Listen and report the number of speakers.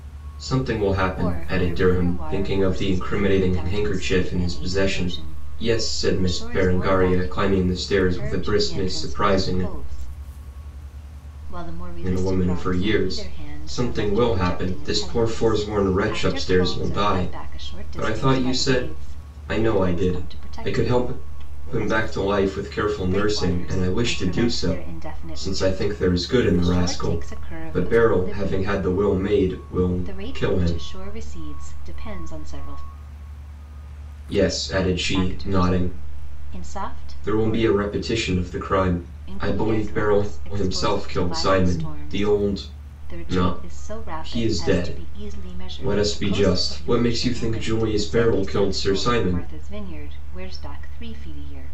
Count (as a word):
two